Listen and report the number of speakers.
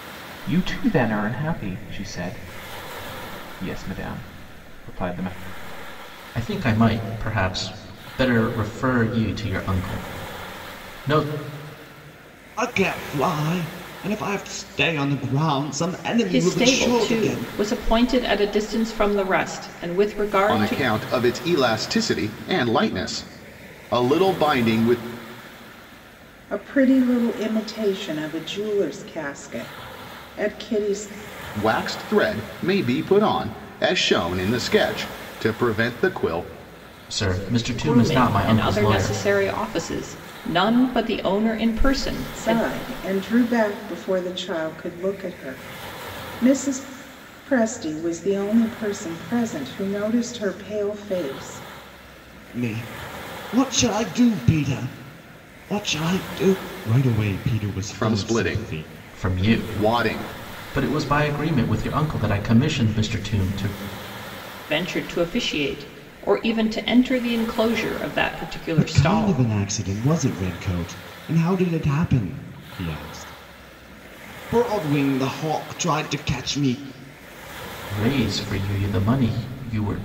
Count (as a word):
six